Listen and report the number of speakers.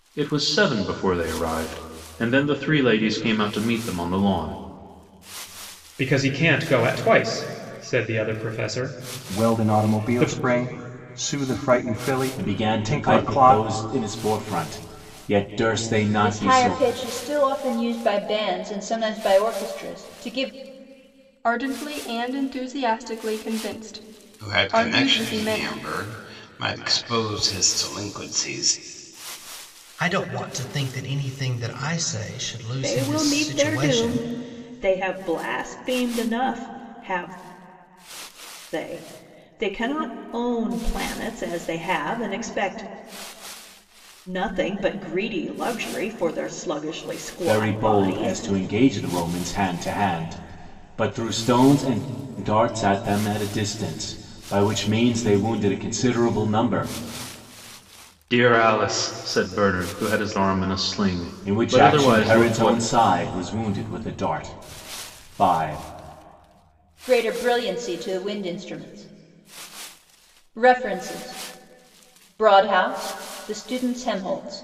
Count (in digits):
9